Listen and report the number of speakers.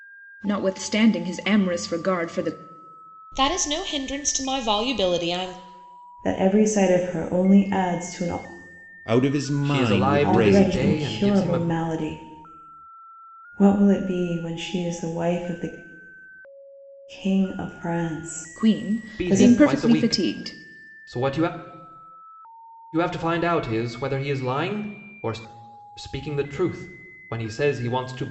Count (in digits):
5